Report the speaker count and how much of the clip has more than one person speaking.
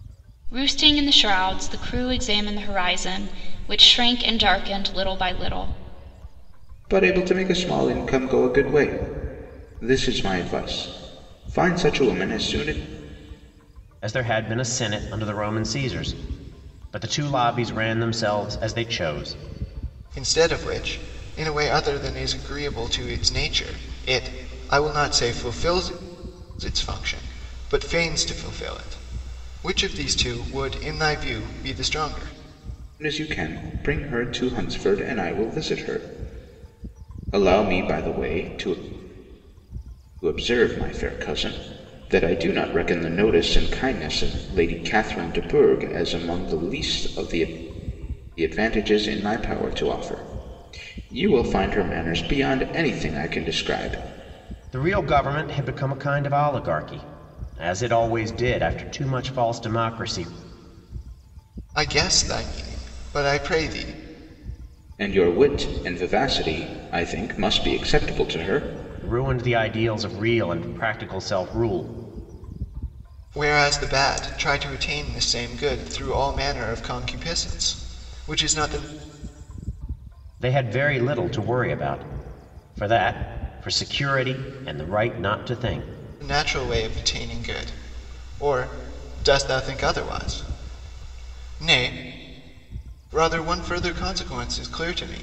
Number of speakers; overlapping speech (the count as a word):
four, no overlap